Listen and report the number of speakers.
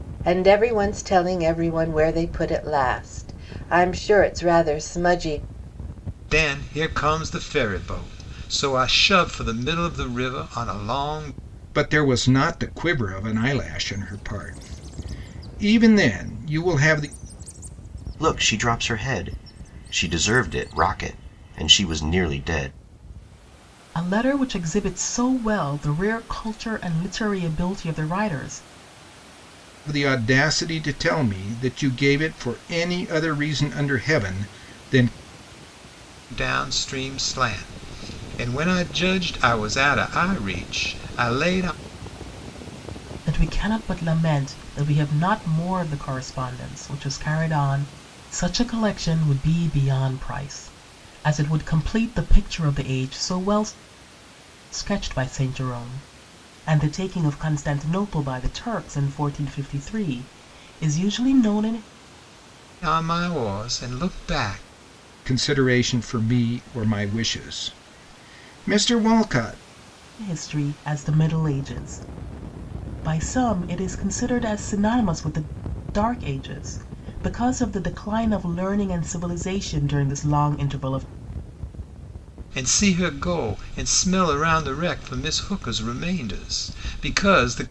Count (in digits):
5